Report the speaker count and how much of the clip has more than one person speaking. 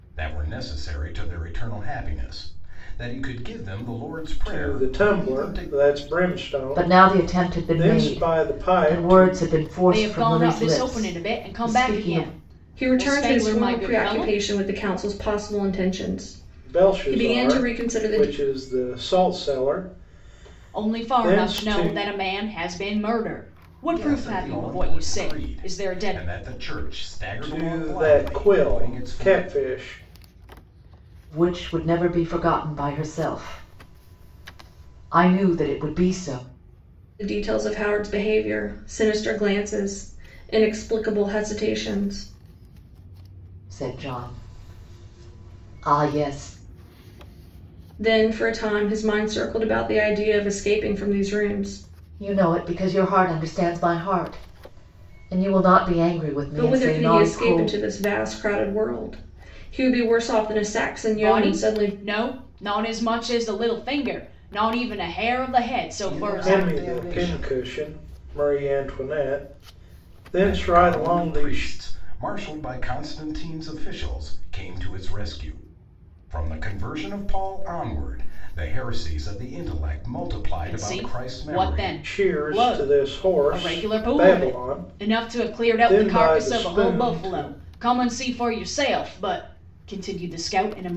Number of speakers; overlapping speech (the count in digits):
5, about 29%